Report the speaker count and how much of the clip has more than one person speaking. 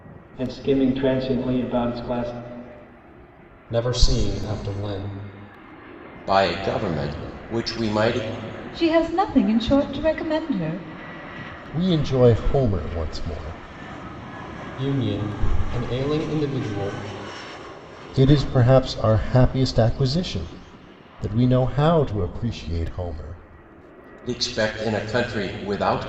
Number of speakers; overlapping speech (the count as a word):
five, no overlap